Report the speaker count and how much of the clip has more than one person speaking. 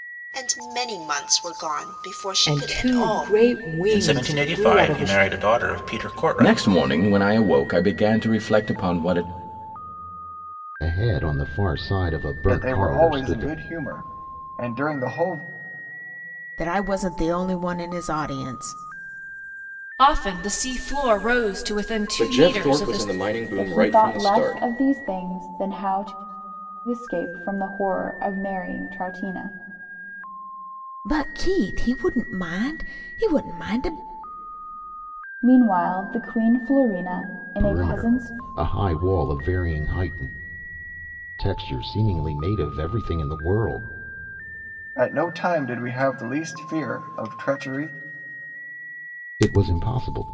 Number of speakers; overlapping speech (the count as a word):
ten, about 13%